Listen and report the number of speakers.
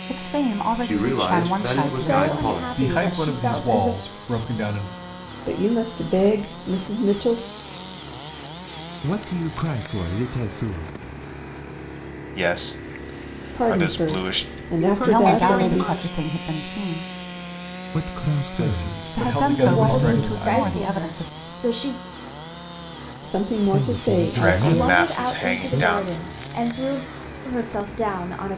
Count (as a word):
seven